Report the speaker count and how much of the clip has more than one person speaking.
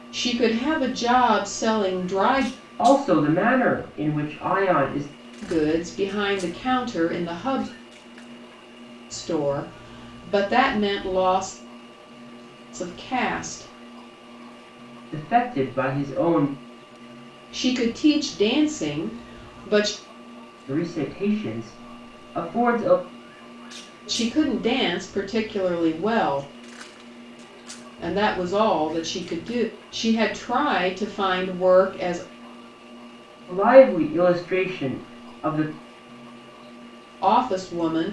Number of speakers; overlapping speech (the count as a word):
two, no overlap